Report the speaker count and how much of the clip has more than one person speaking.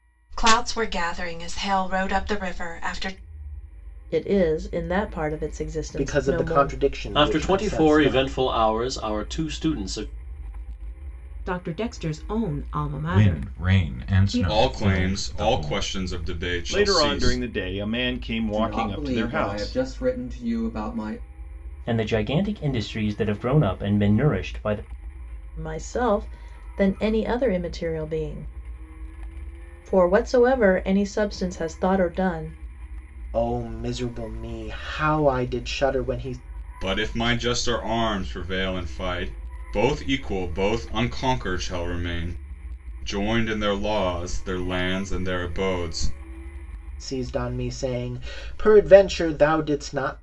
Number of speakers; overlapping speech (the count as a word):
ten, about 14%